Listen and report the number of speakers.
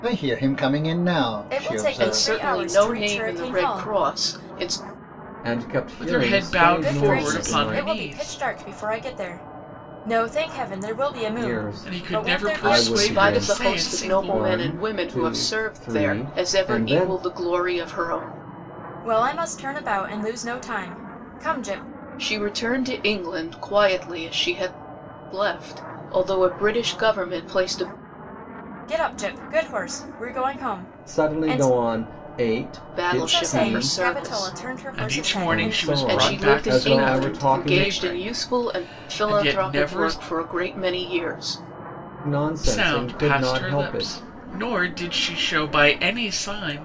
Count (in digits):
5